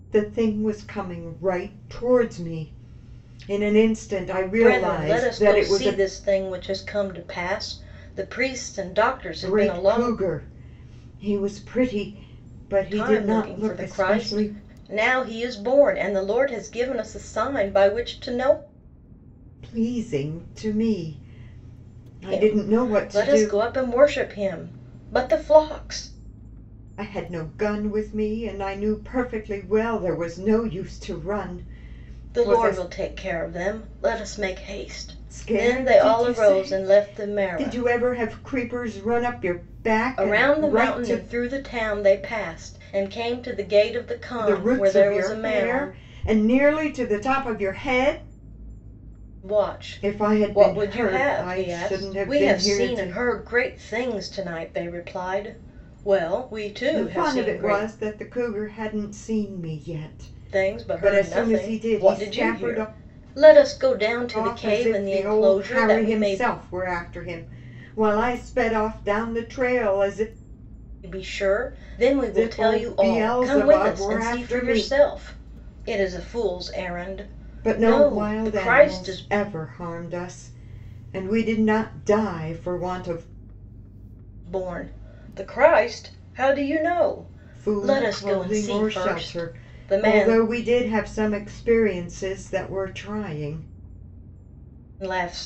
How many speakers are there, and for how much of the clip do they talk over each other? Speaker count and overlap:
two, about 28%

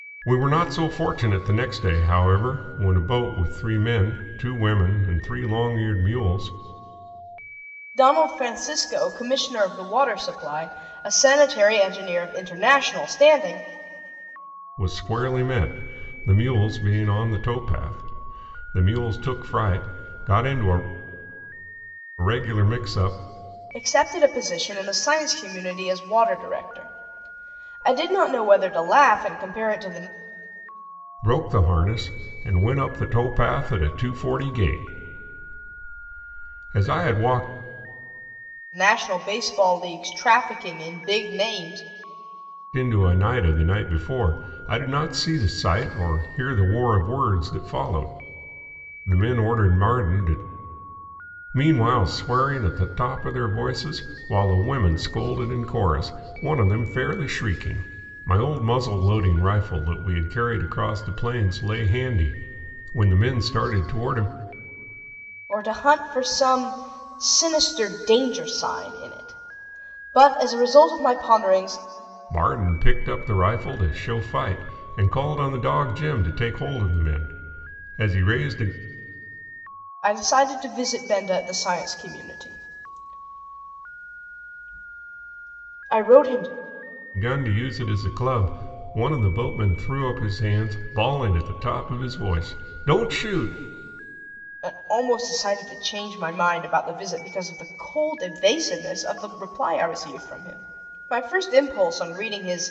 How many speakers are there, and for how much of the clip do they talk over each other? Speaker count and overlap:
two, no overlap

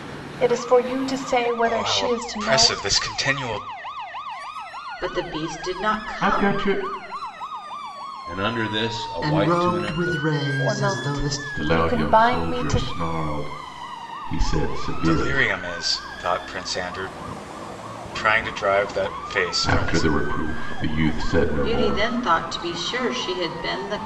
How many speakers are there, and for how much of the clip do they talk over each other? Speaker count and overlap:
six, about 26%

